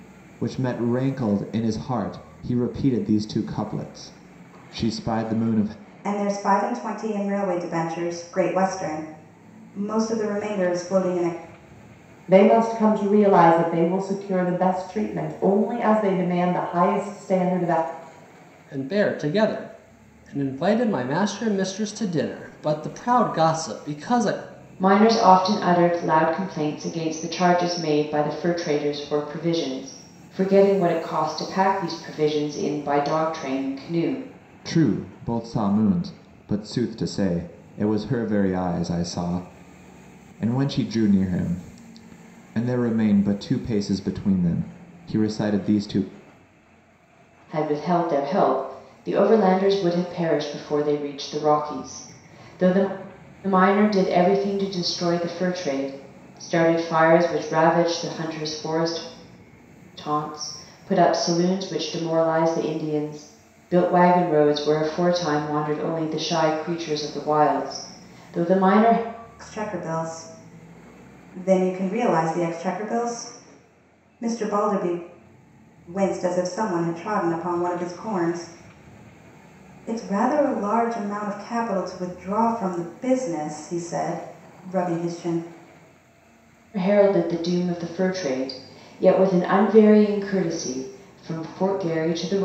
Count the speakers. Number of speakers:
five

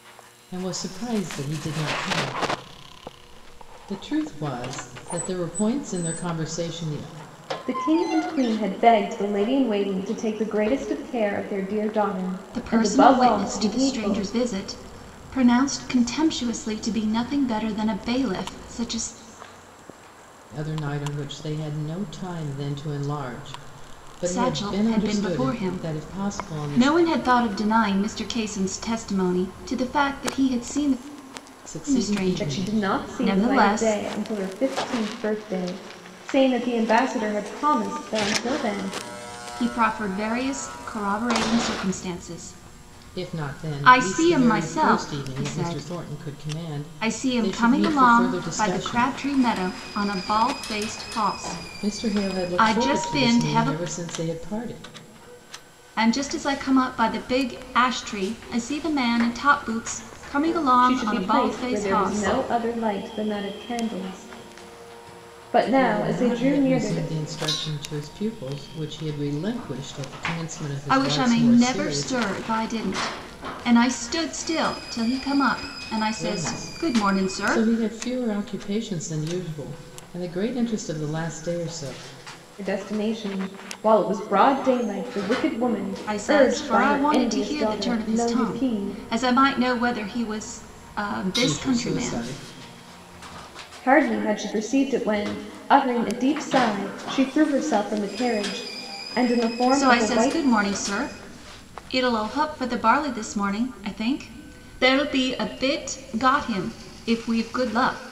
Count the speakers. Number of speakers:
three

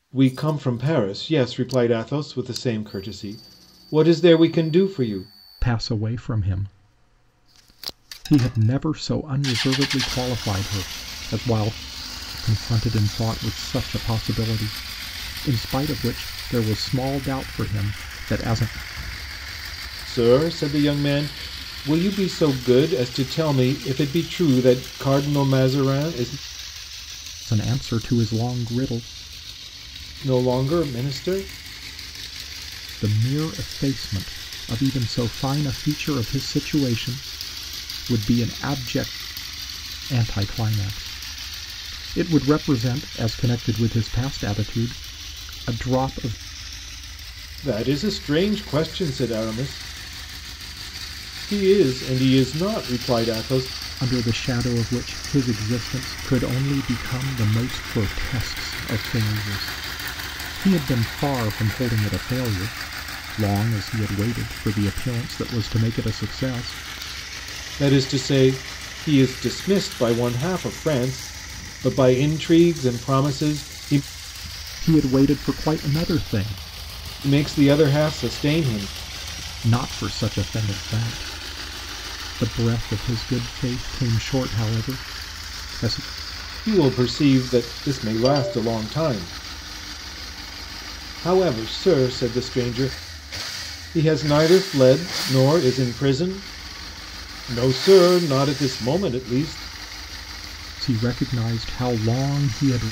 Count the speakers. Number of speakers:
two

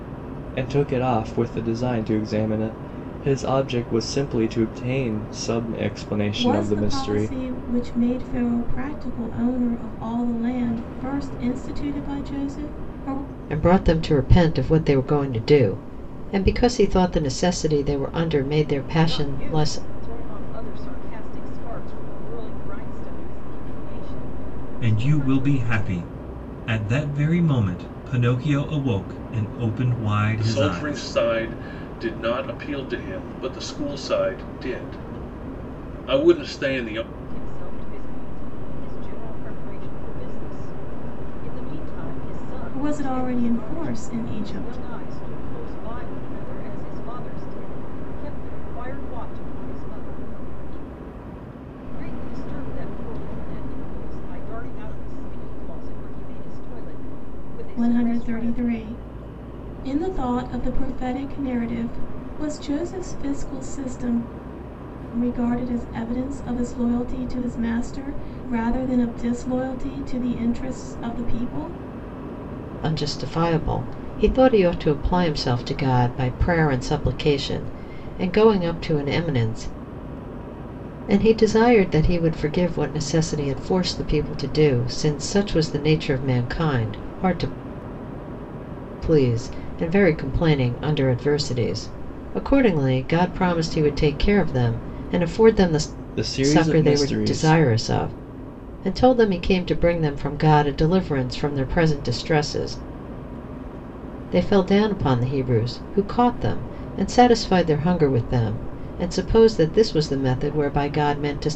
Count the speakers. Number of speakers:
six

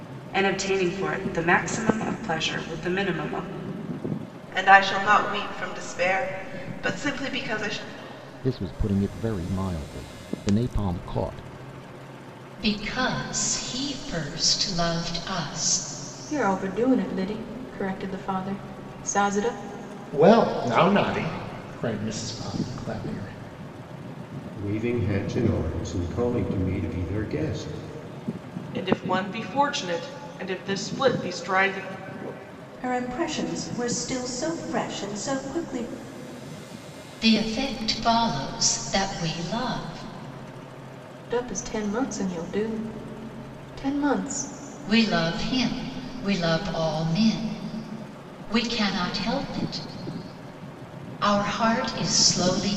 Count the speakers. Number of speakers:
nine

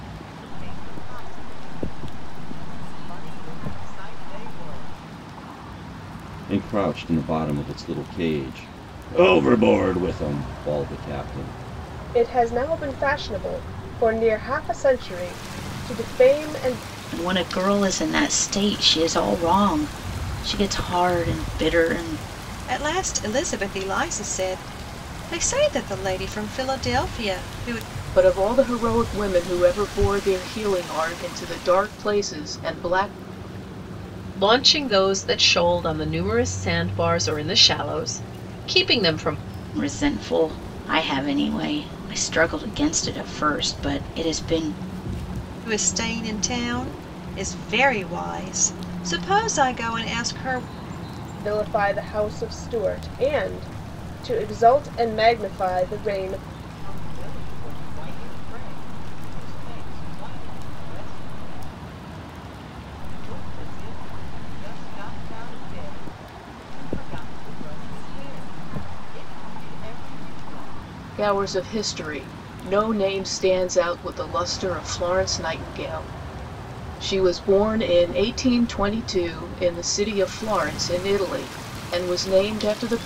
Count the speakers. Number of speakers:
seven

